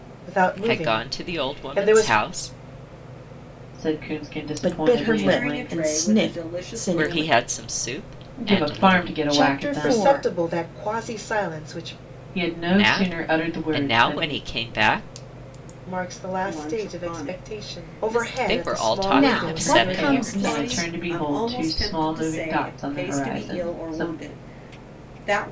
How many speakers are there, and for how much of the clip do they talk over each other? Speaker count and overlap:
5, about 61%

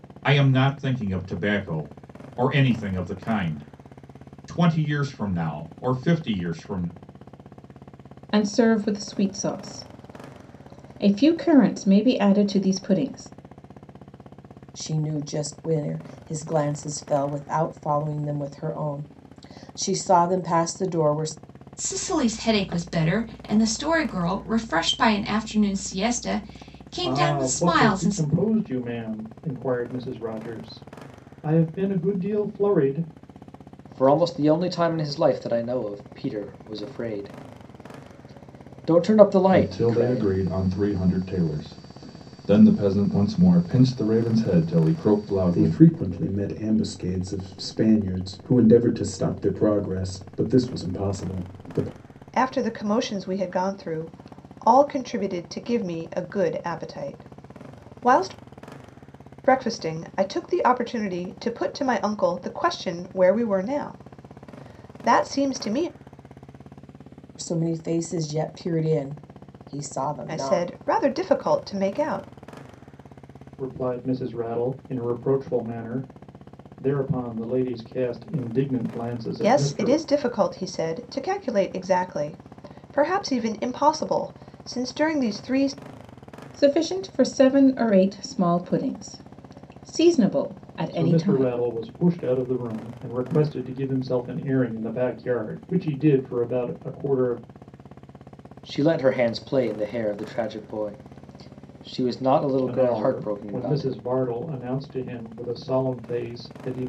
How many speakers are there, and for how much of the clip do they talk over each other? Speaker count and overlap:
9, about 5%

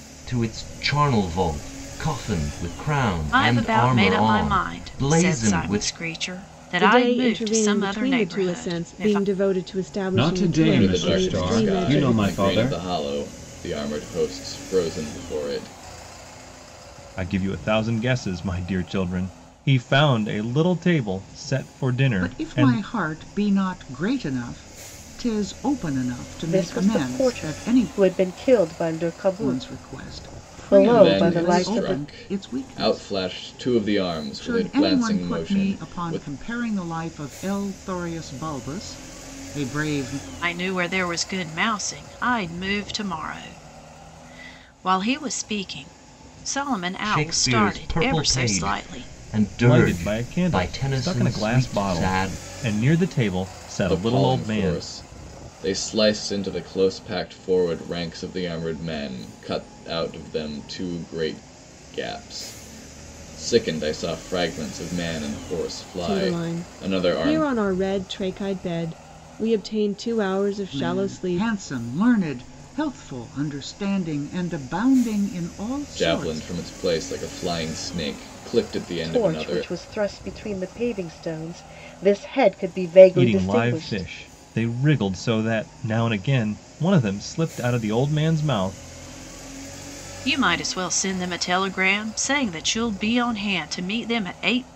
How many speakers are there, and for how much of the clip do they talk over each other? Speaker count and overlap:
8, about 27%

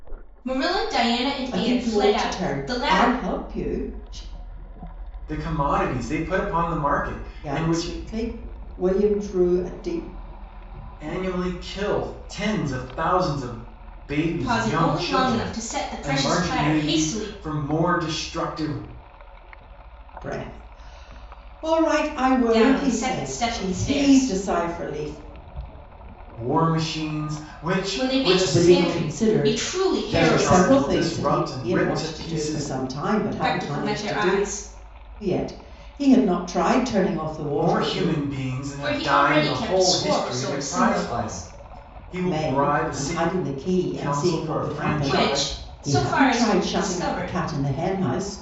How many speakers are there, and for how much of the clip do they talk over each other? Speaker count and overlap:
3, about 41%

